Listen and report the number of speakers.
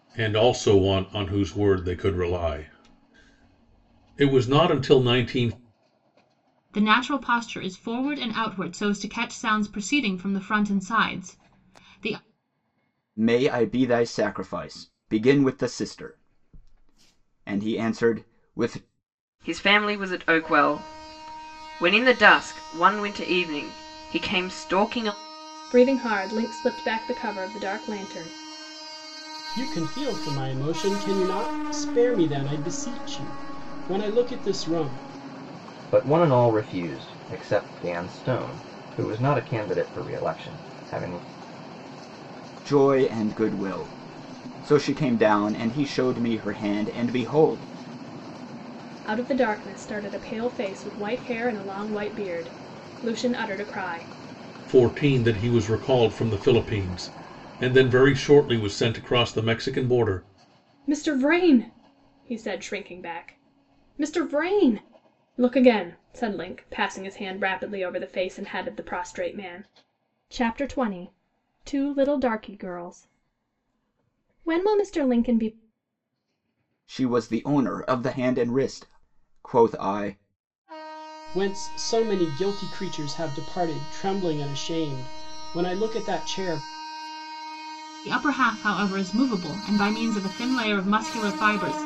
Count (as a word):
seven